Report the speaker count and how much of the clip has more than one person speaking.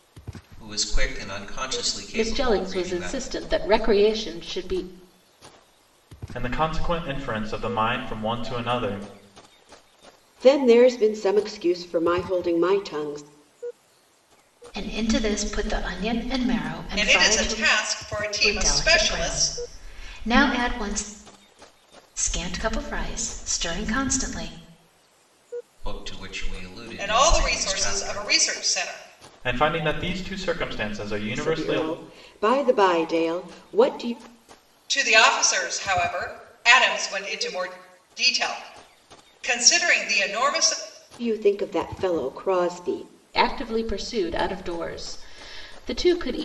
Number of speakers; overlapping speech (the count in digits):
6, about 10%